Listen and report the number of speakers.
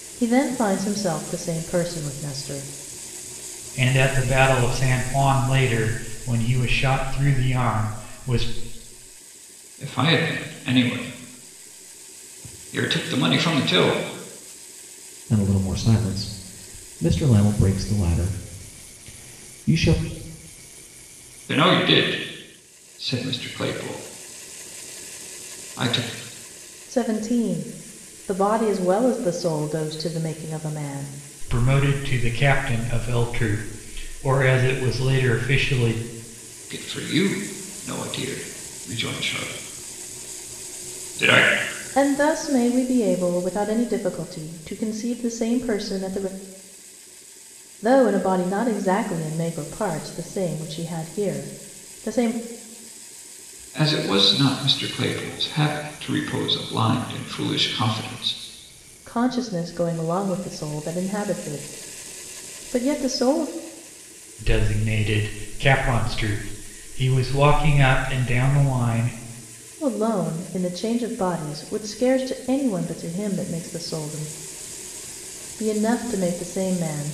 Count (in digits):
4